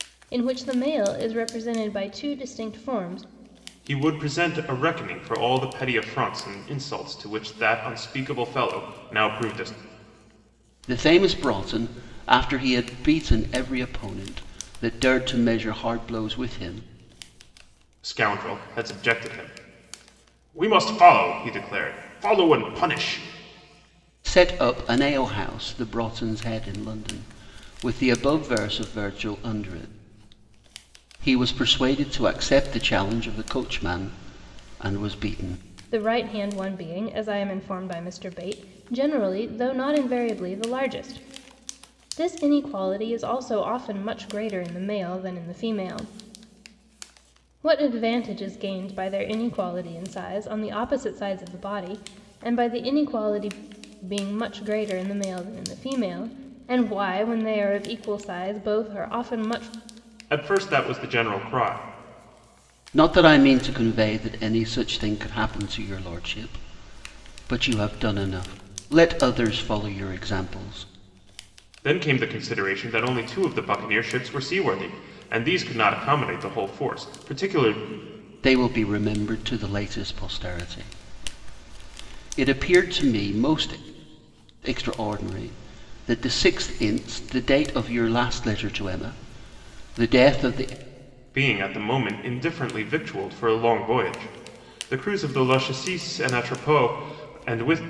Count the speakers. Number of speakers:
3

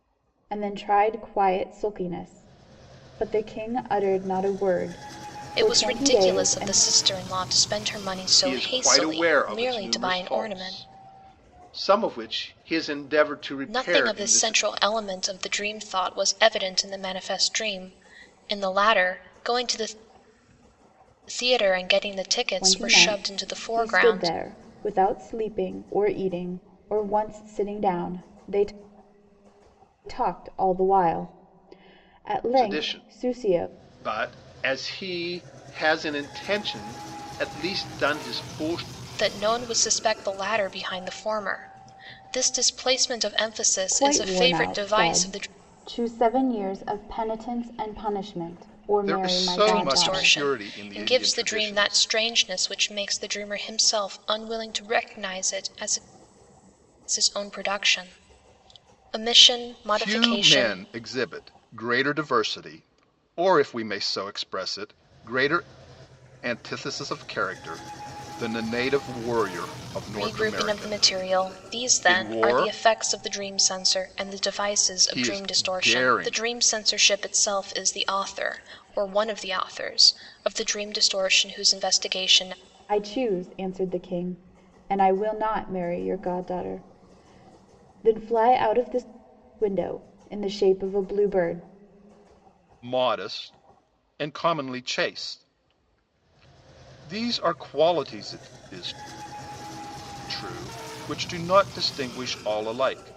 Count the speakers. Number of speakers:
3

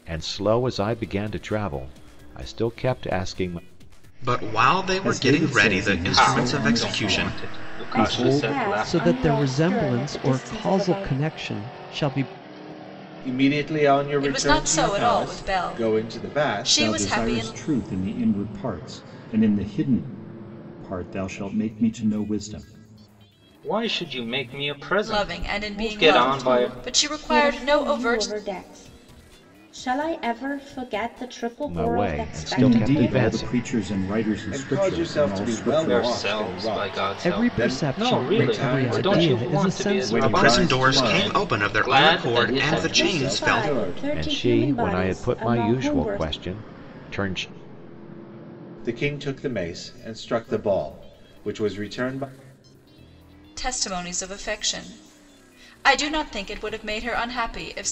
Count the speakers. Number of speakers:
8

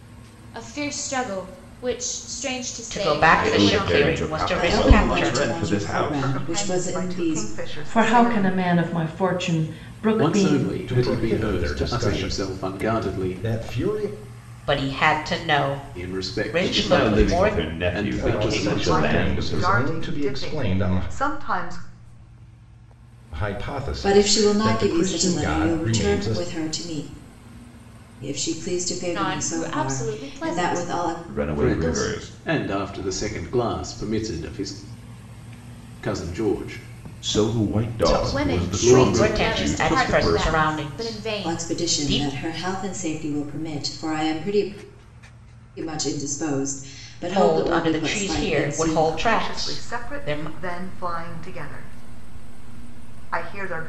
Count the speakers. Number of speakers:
8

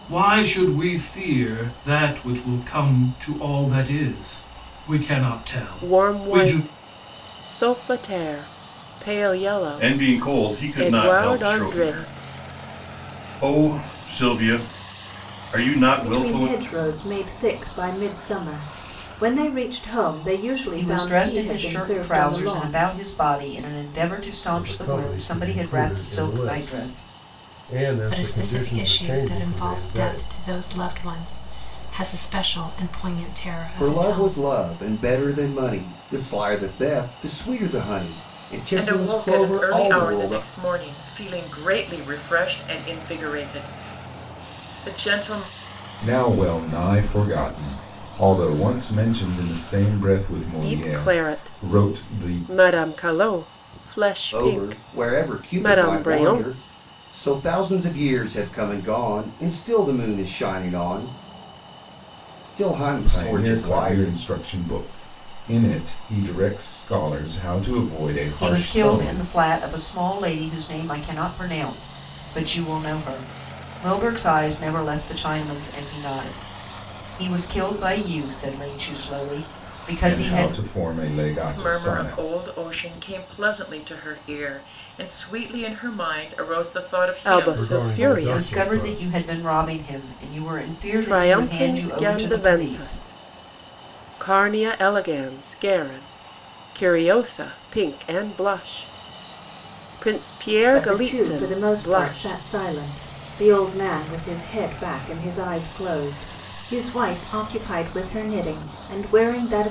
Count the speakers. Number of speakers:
10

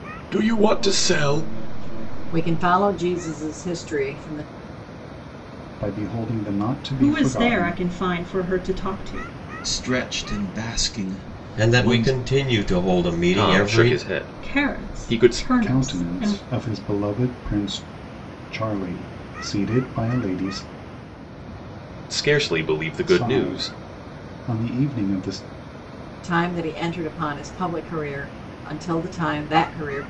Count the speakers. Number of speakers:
7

